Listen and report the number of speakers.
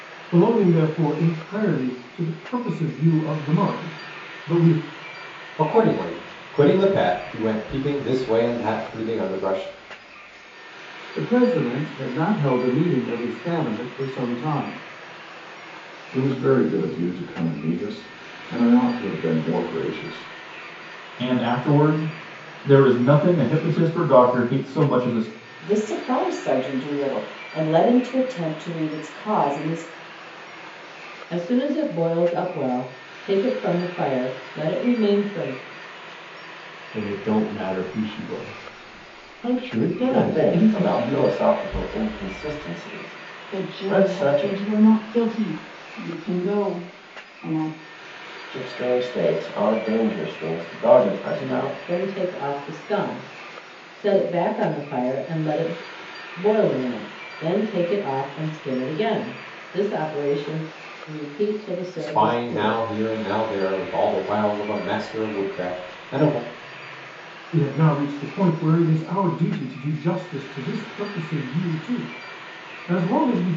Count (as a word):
ten